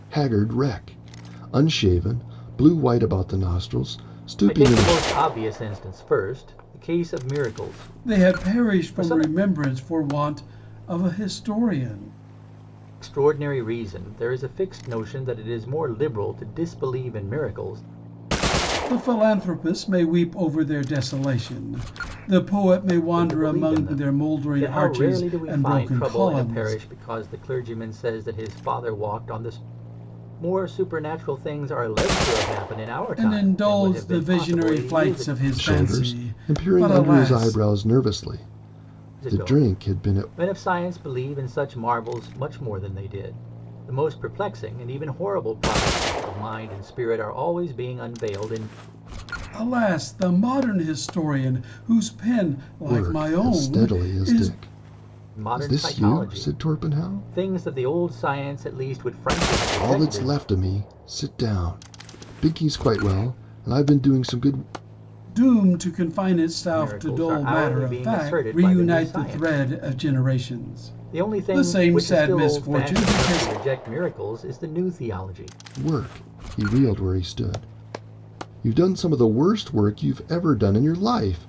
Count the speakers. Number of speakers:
3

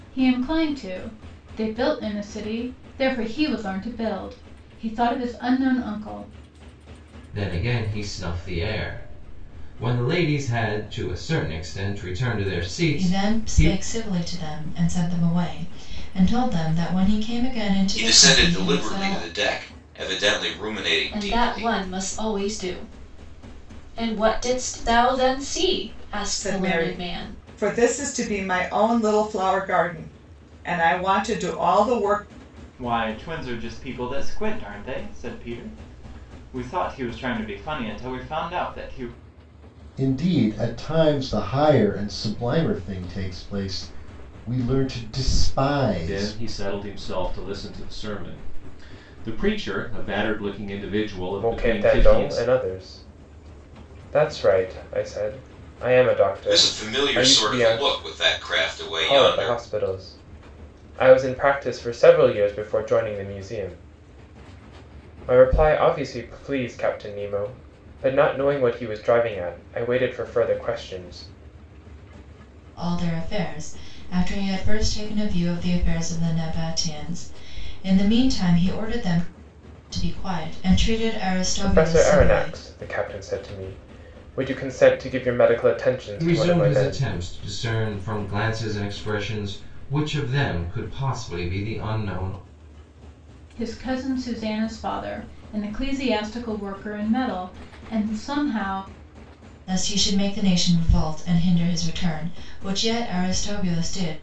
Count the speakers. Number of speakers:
10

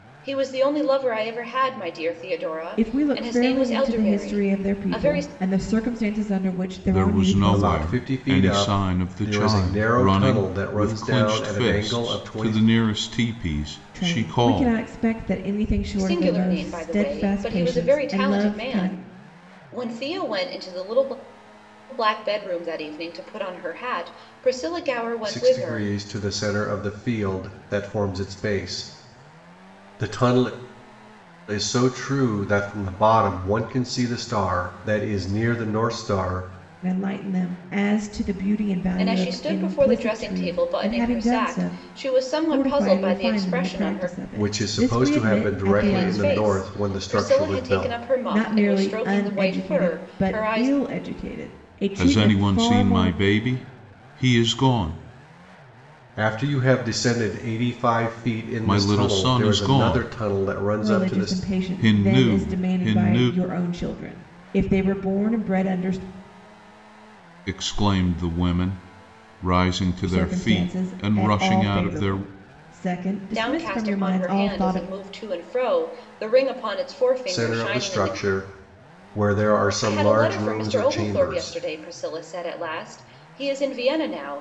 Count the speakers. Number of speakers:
4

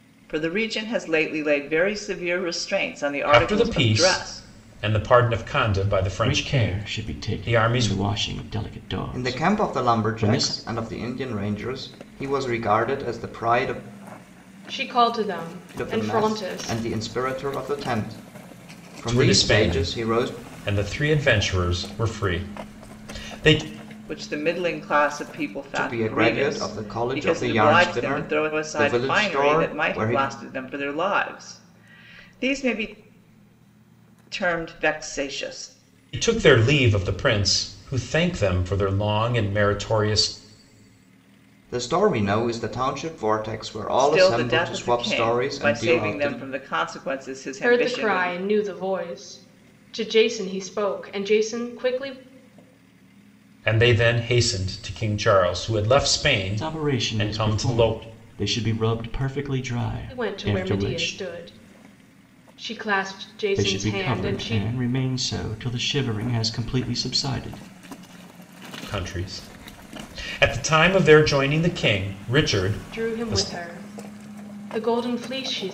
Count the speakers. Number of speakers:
5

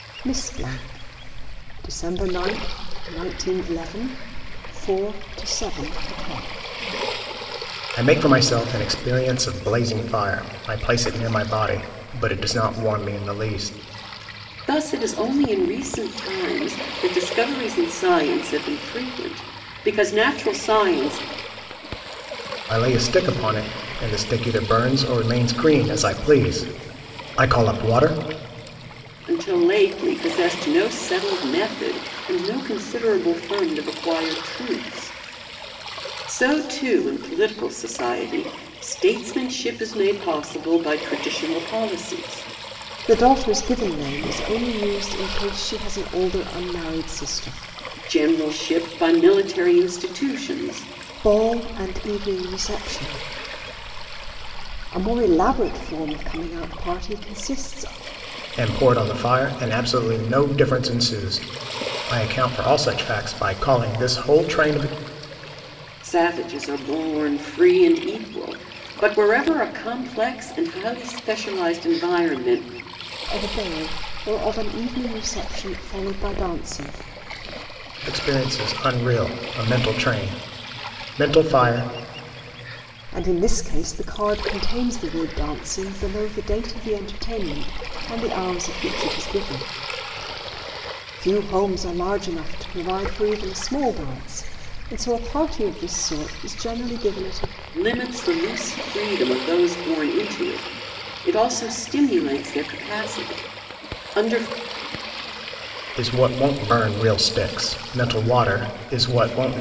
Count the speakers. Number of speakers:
3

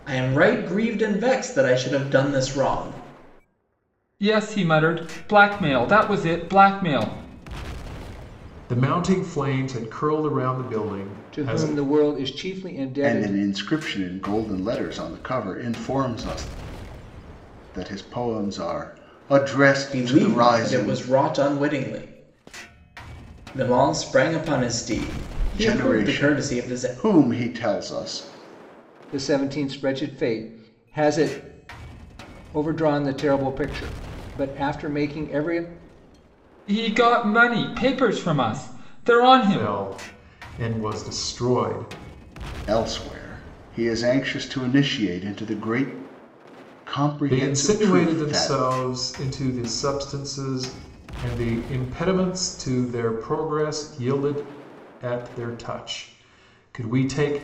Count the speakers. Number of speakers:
5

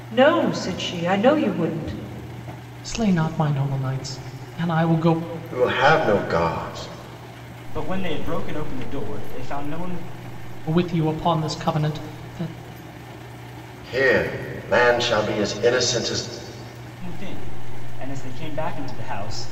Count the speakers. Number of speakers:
4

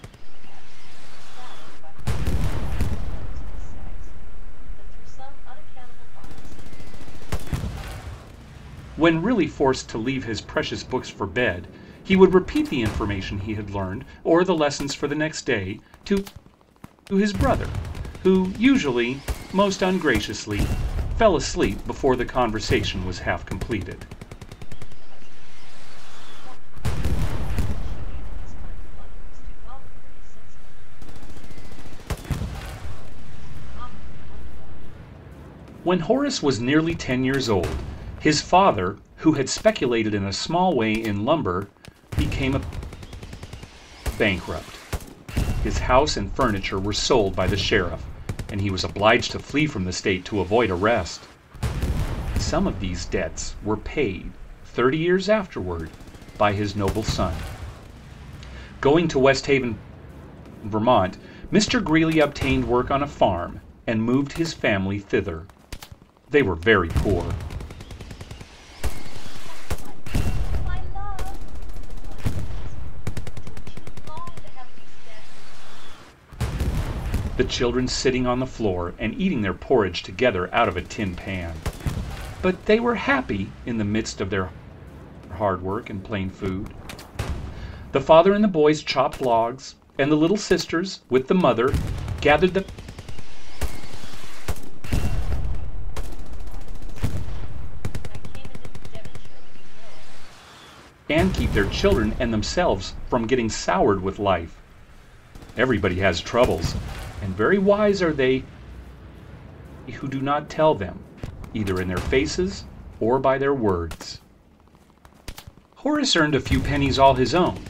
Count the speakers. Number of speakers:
2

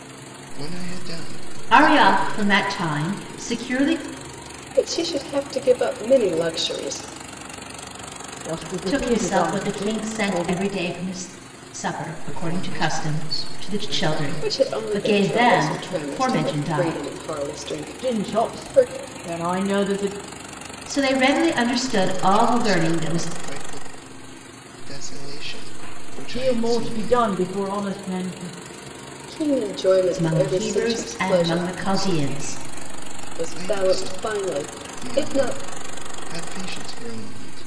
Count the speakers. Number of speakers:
4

